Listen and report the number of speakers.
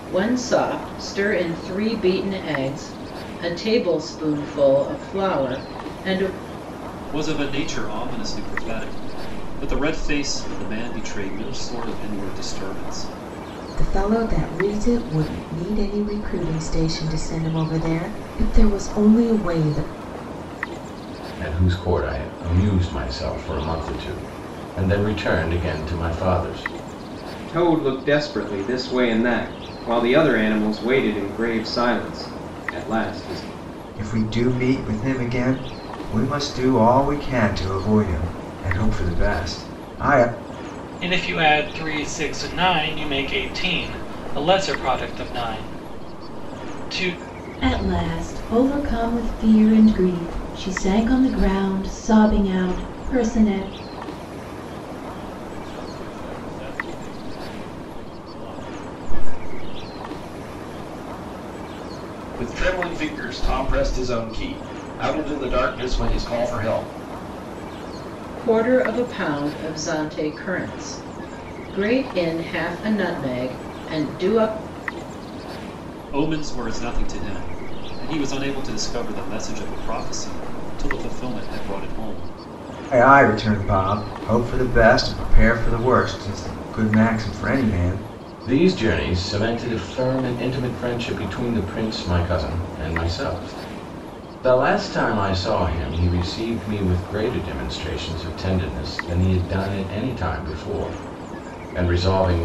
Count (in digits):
10